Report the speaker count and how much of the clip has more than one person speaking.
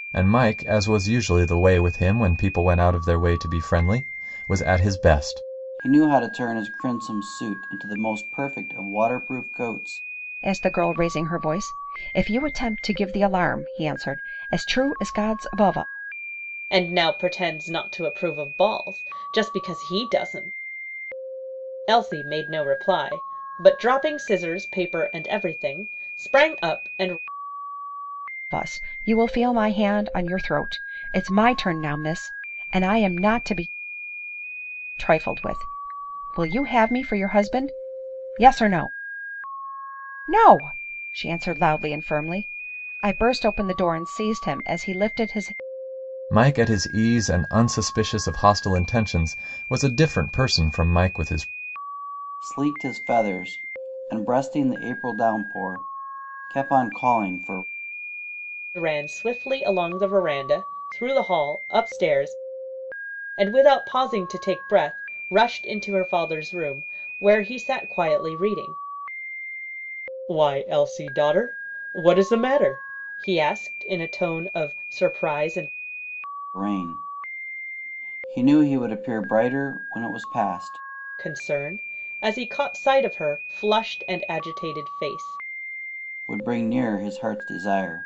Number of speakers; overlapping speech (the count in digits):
4, no overlap